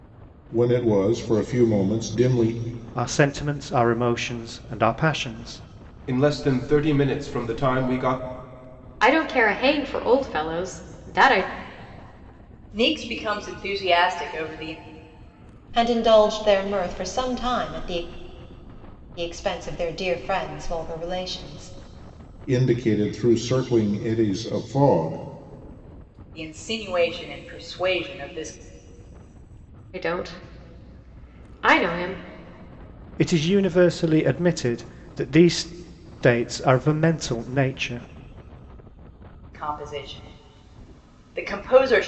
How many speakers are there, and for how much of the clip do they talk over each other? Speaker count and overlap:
6, no overlap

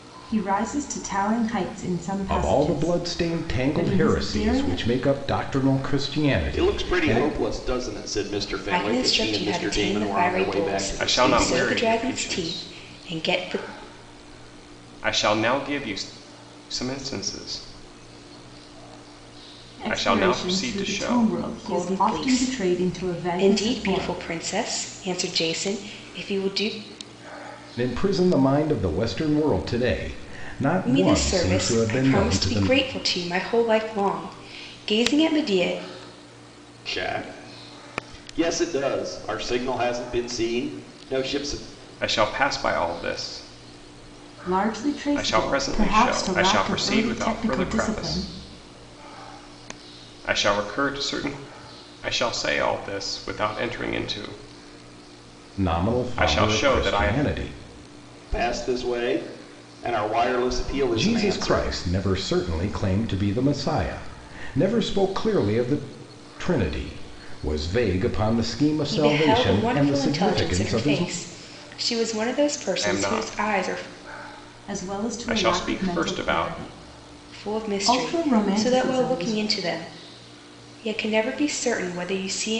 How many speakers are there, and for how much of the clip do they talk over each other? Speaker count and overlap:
5, about 34%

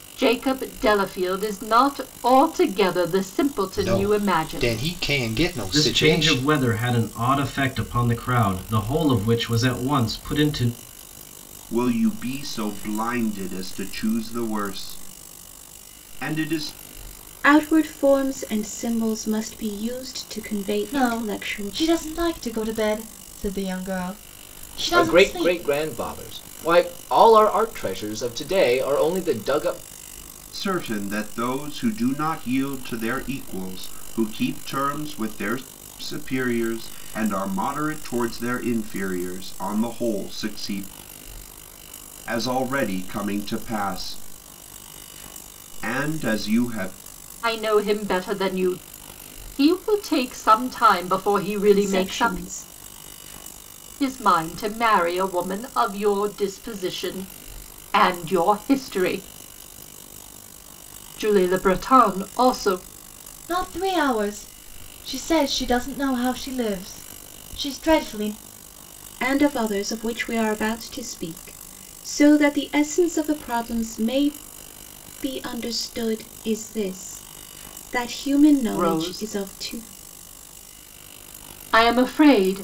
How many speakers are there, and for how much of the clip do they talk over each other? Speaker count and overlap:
7, about 7%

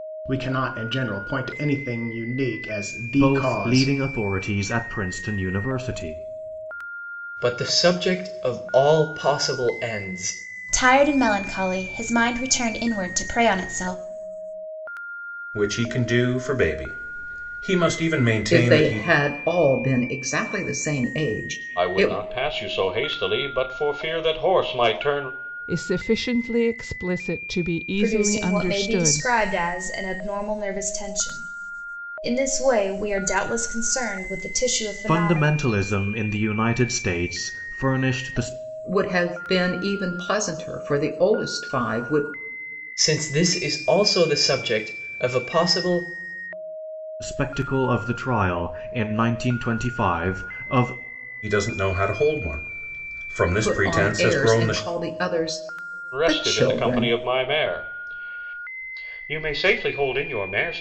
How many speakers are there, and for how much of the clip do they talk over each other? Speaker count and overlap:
9, about 10%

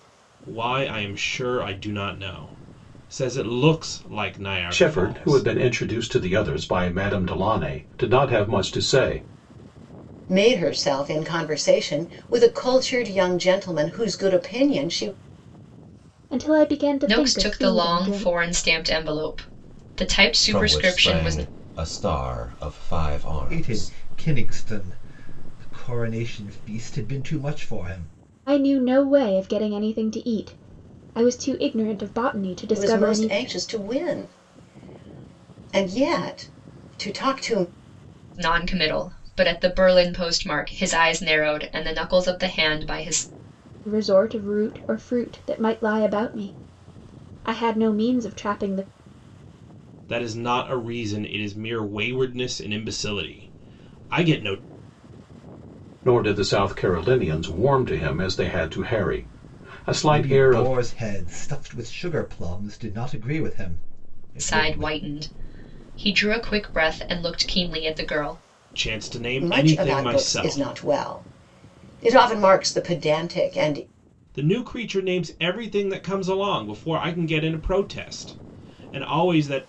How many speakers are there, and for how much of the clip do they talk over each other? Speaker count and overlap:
7, about 9%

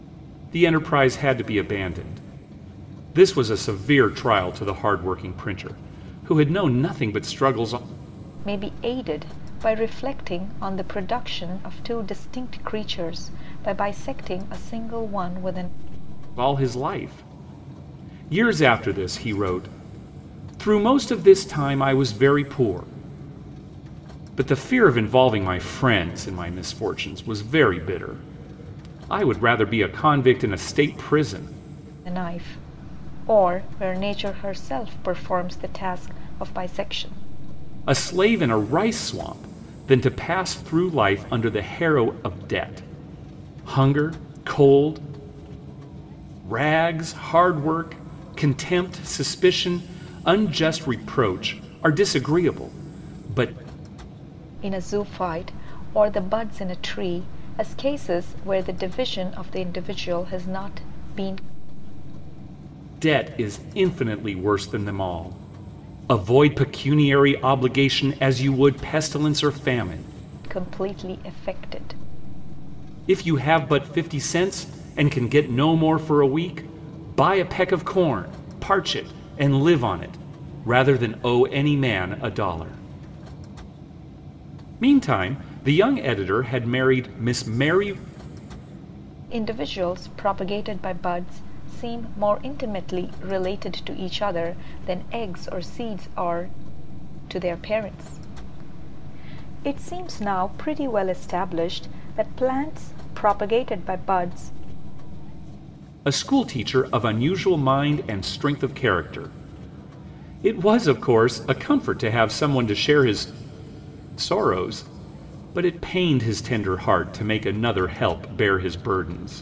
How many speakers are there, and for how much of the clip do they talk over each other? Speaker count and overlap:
2, no overlap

